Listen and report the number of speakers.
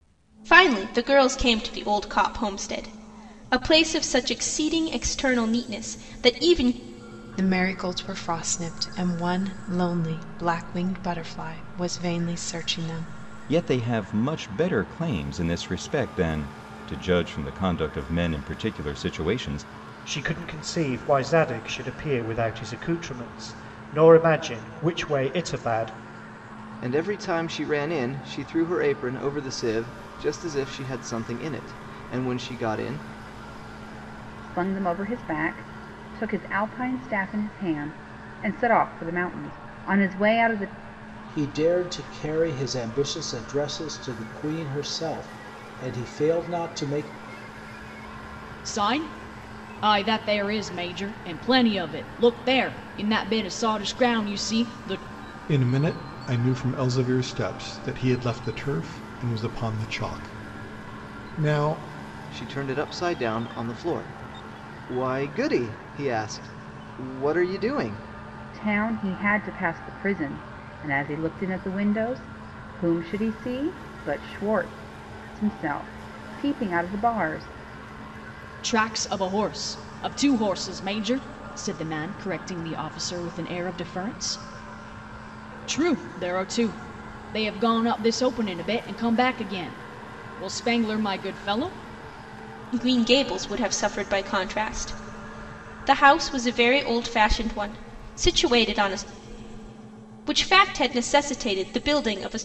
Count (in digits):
9